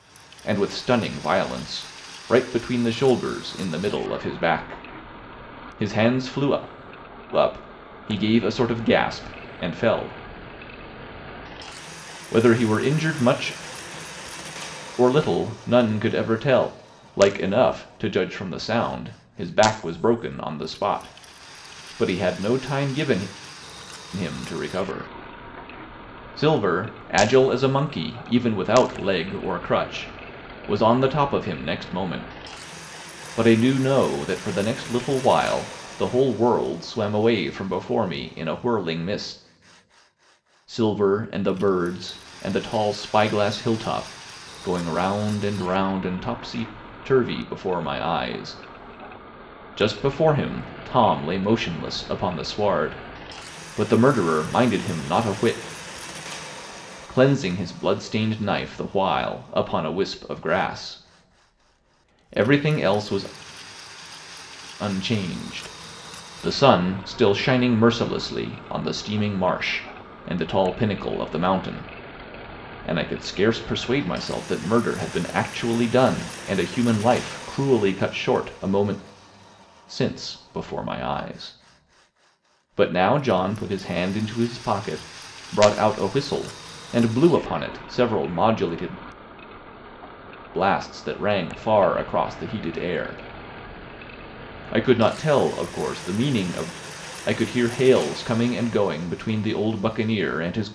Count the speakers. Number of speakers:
1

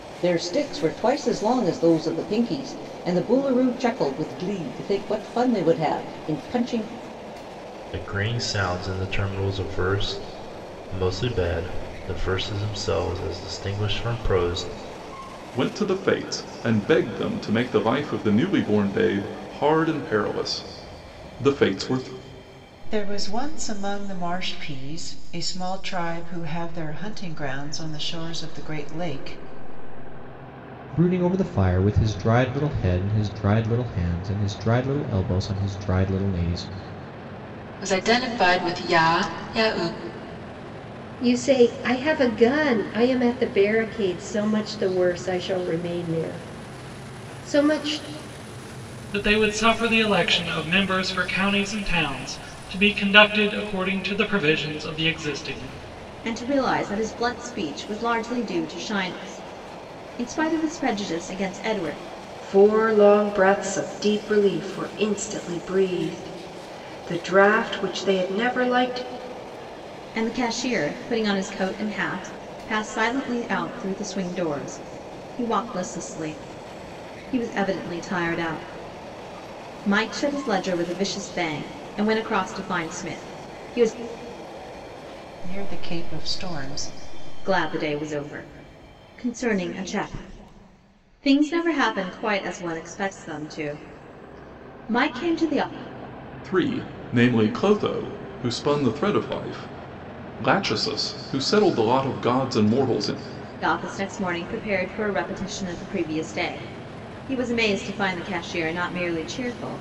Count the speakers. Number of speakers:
10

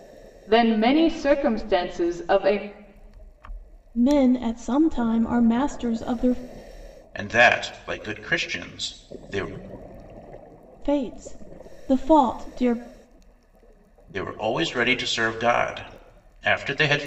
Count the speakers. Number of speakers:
3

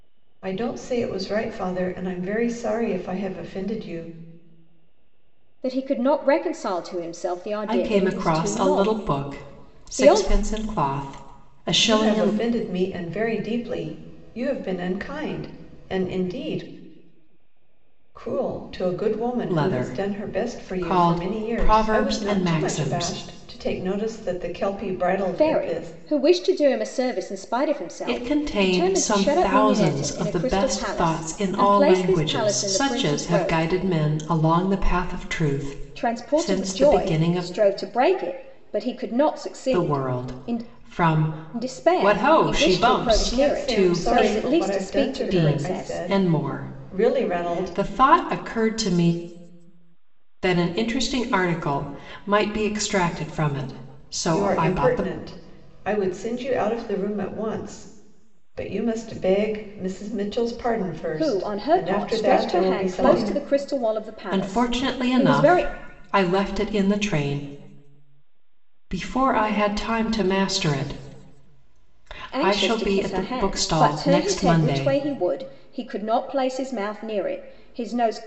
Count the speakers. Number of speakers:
3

